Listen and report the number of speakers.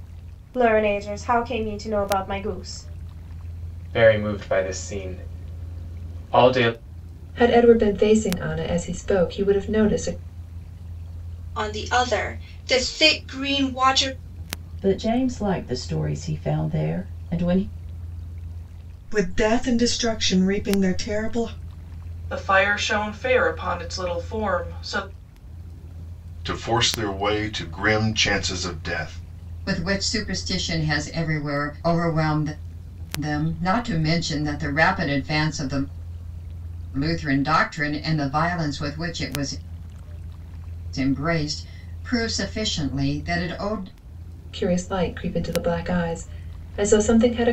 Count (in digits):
9